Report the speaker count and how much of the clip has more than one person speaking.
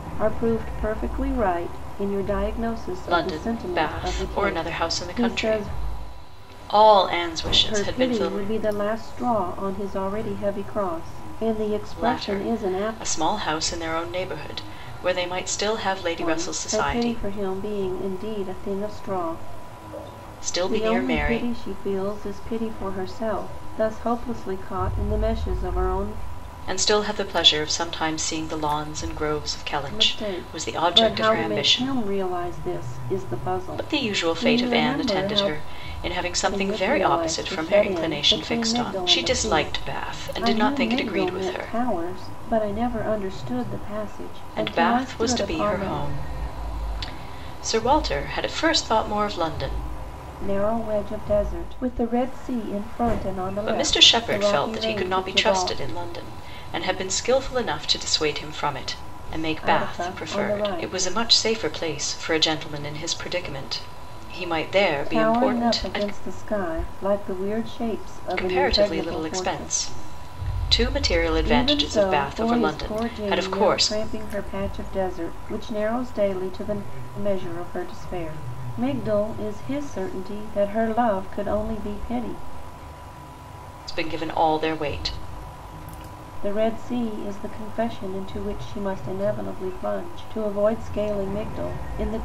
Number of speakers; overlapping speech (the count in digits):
2, about 28%